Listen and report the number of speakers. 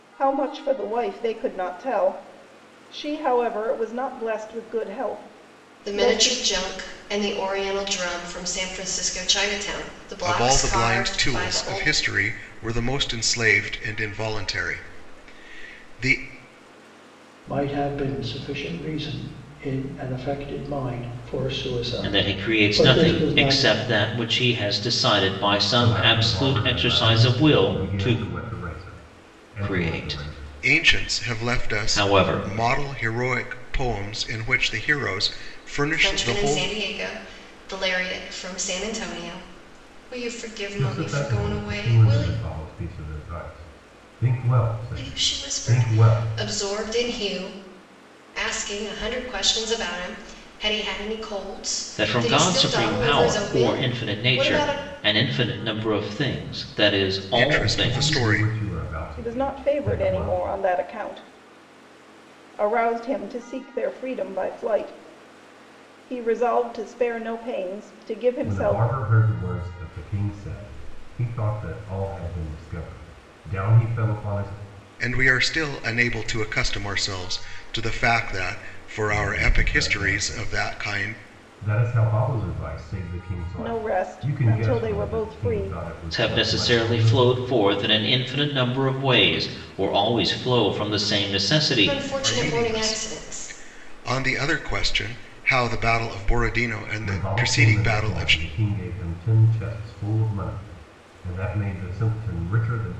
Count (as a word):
six